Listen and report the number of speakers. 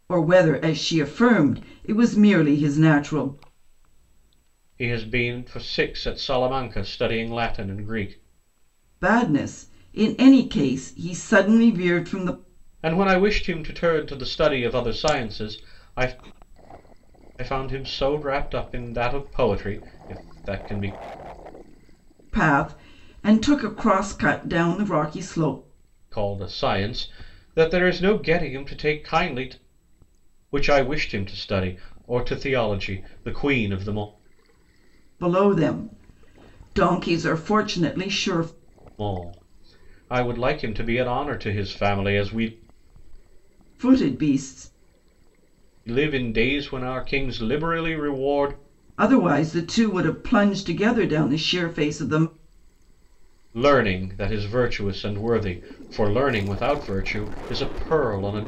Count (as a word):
two